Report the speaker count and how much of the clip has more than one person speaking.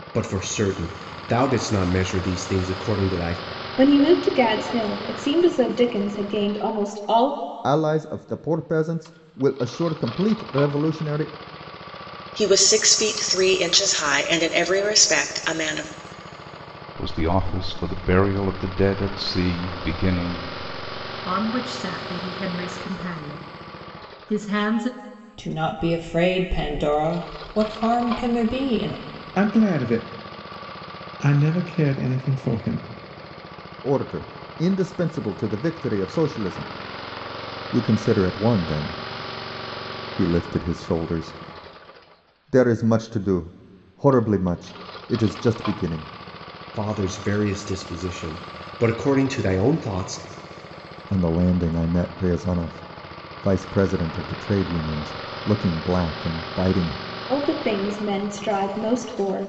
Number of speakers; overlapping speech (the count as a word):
eight, no overlap